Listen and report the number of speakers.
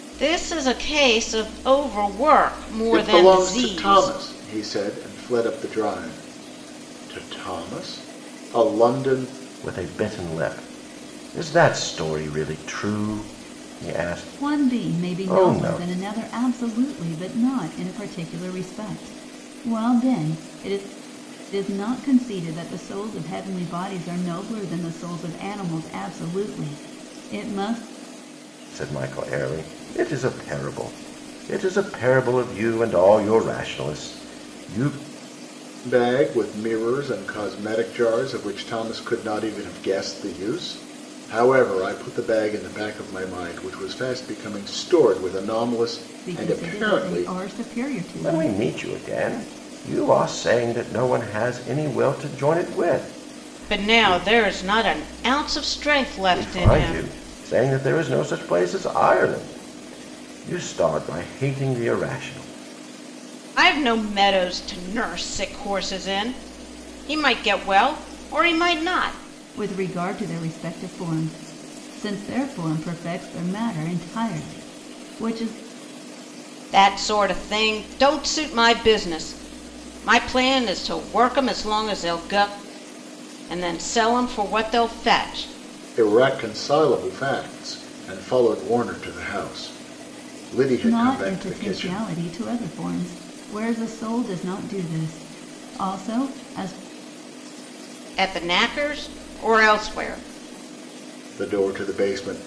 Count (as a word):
four